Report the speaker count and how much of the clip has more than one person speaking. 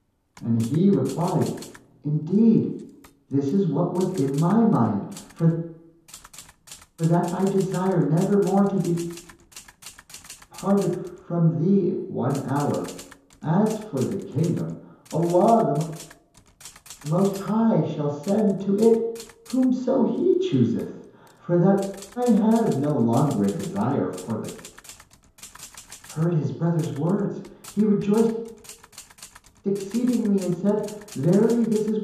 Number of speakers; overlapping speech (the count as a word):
one, no overlap